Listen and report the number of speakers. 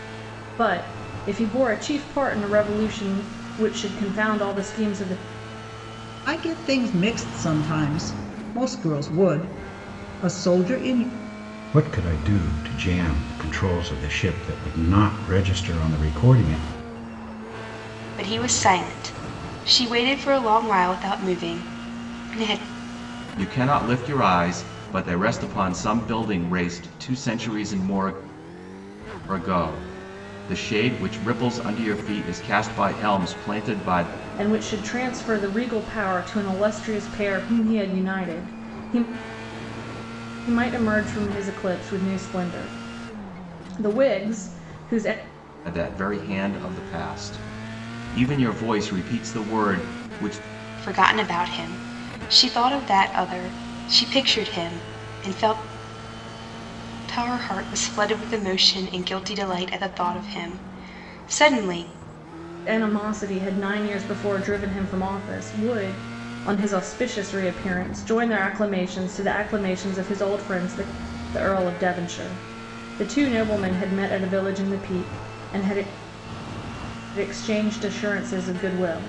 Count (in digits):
5